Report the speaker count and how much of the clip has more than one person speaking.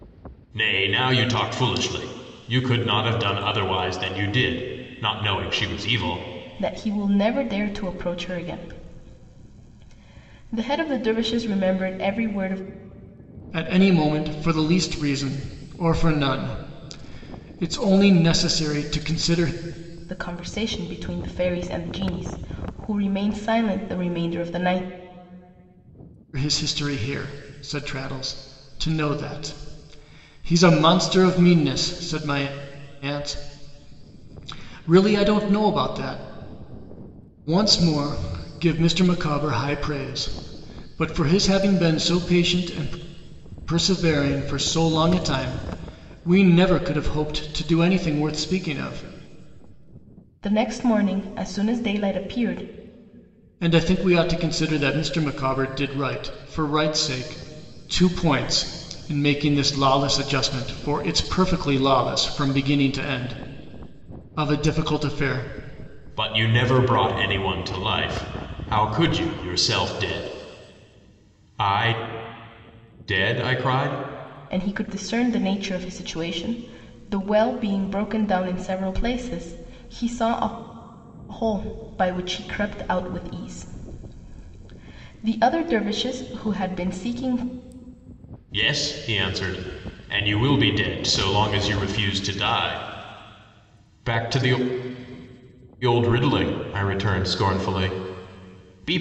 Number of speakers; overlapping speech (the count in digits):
3, no overlap